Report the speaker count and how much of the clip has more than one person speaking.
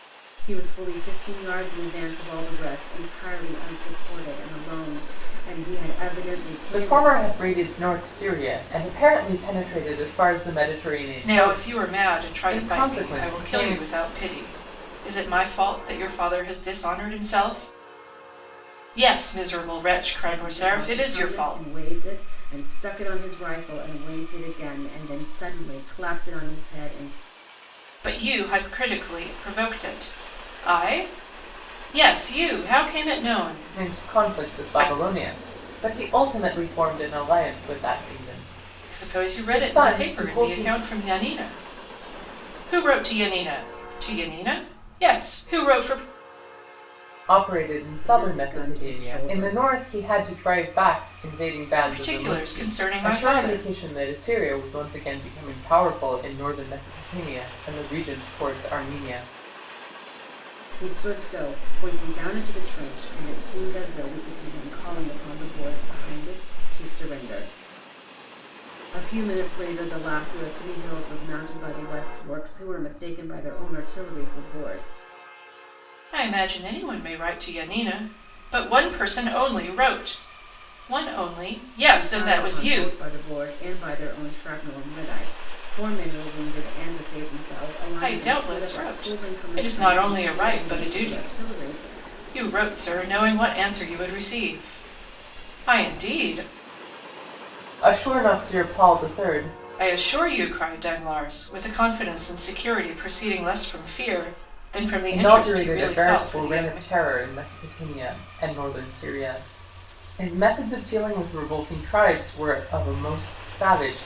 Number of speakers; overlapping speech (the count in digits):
3, about 15%